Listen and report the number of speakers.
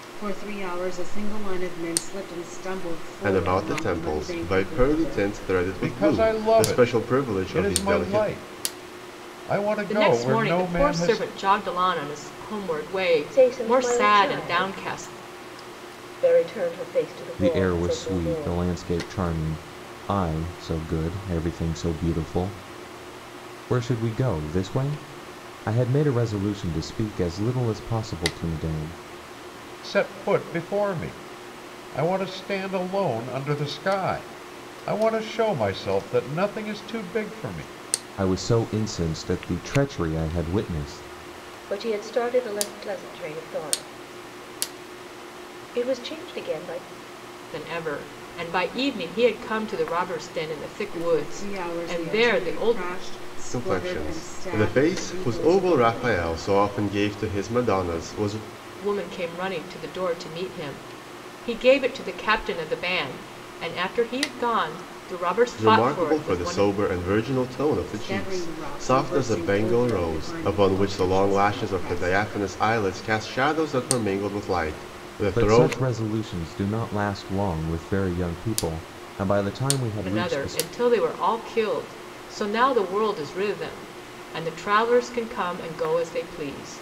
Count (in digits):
6